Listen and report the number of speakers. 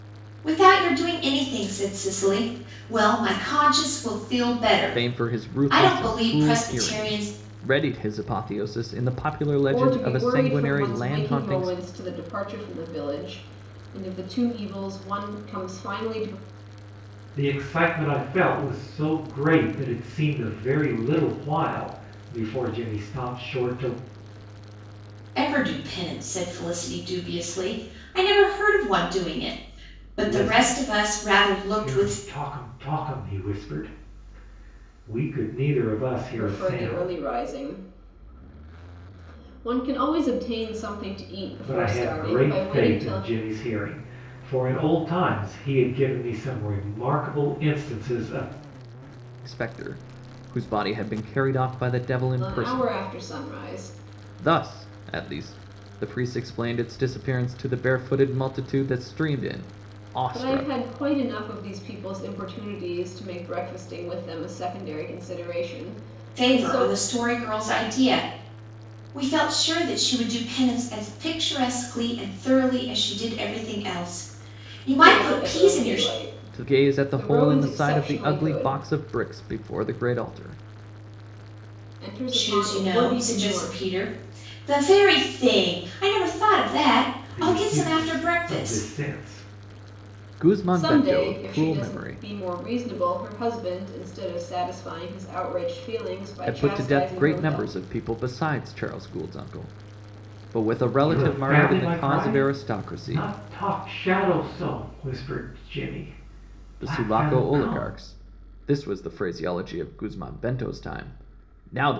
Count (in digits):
4